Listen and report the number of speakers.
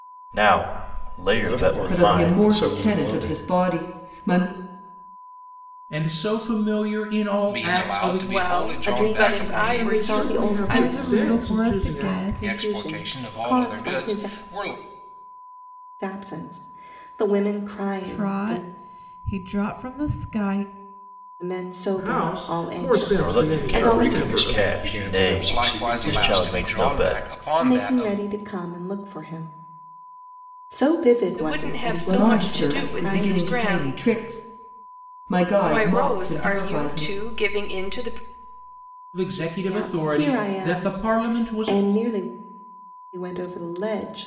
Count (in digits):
9